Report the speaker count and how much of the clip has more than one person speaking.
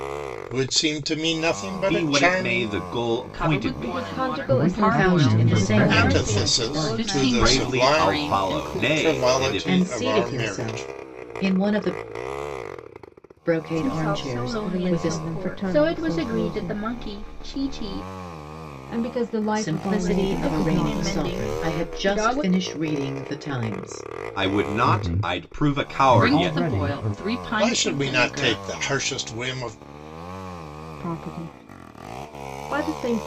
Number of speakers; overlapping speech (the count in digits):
7, about 54%